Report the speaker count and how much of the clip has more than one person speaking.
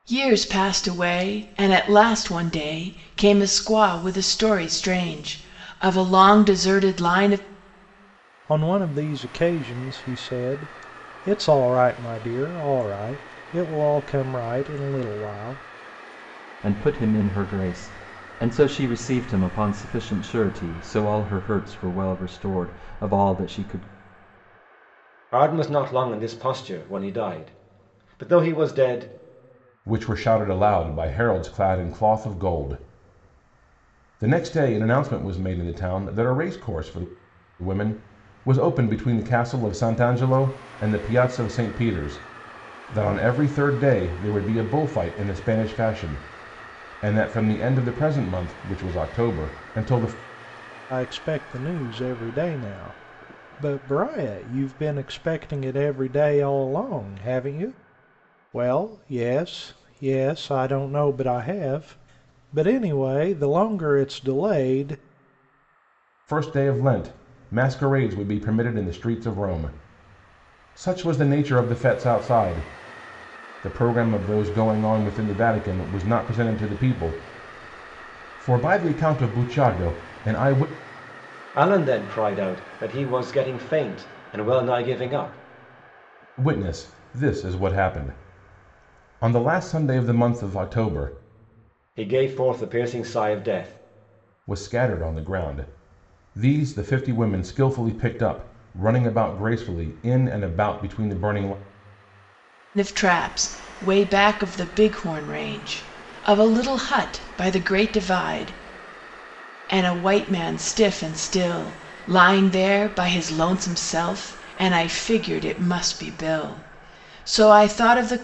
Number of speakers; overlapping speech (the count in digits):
5, no overlap